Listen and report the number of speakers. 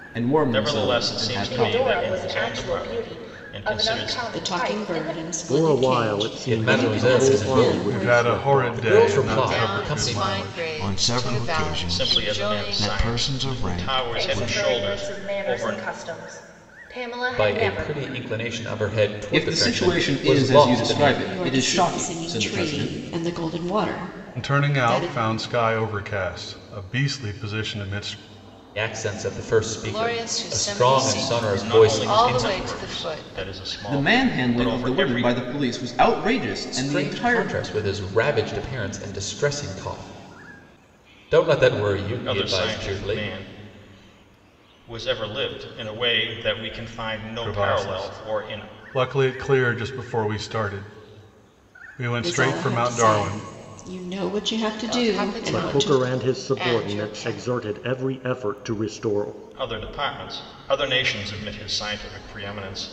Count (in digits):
9